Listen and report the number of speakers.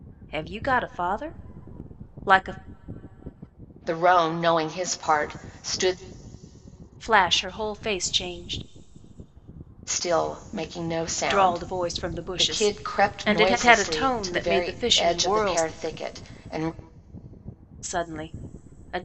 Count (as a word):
two